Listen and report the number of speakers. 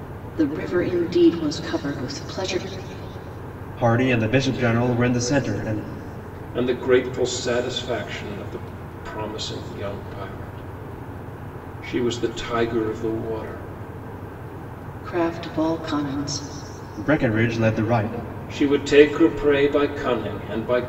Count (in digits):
3